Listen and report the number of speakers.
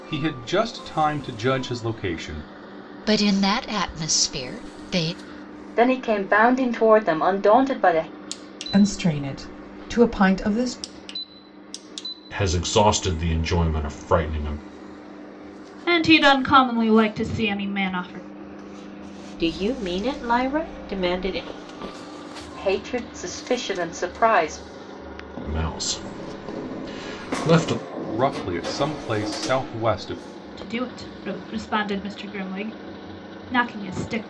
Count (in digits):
7